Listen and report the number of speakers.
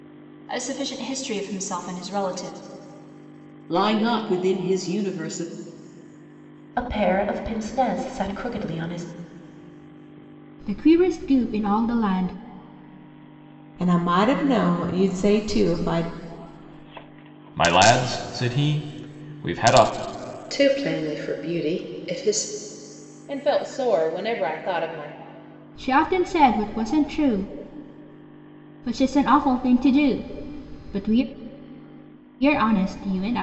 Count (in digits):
8